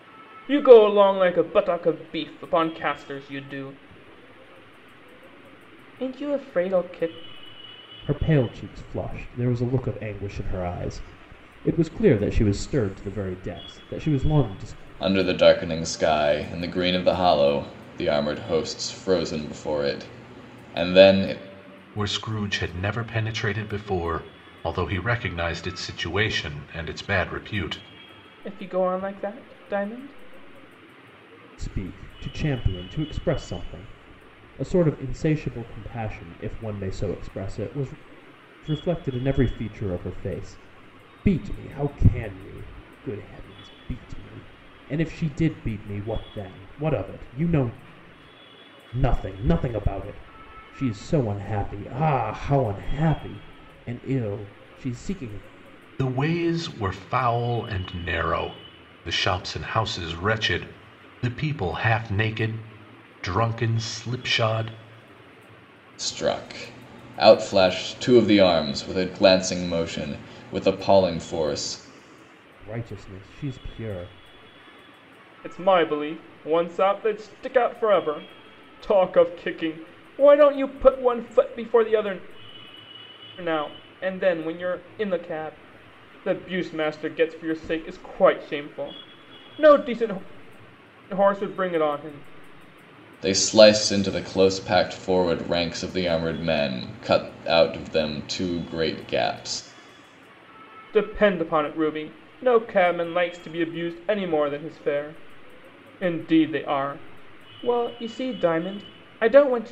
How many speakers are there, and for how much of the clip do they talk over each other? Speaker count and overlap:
4, no overlap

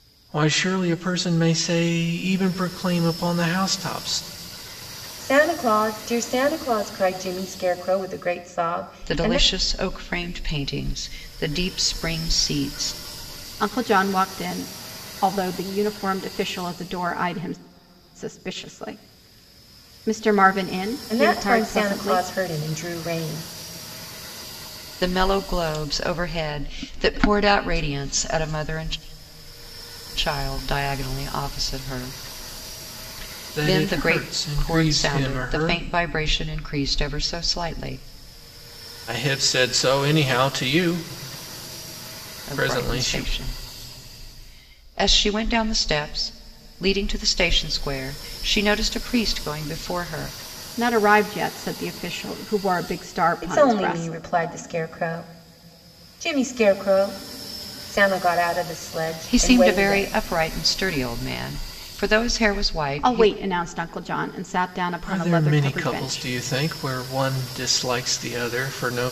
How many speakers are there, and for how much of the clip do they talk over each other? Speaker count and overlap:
4, about 12%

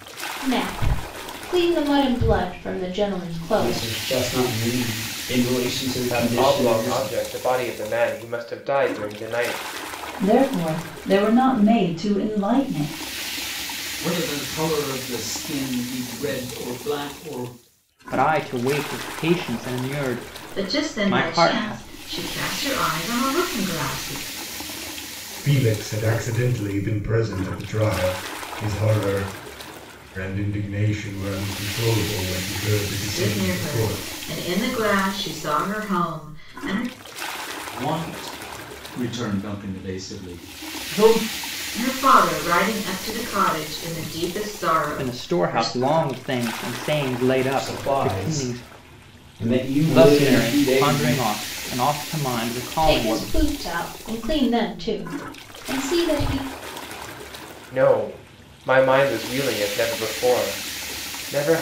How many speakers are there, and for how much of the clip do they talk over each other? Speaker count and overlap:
8, about 13%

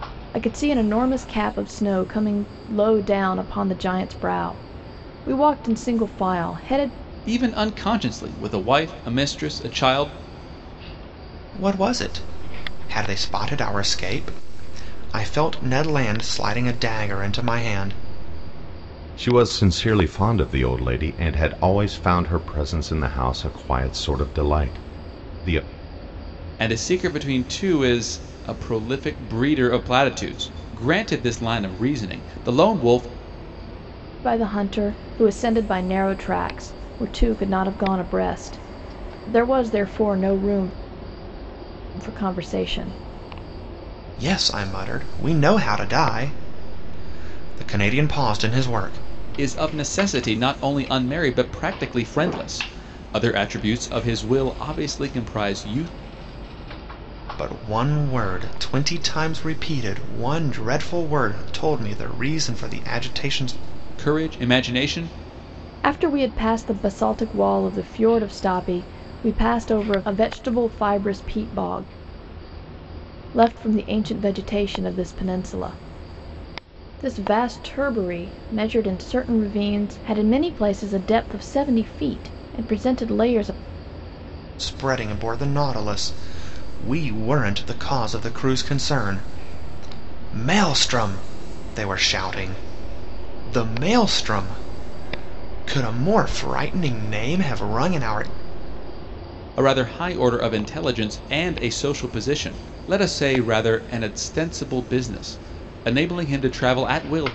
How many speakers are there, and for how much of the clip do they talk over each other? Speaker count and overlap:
4, no overlap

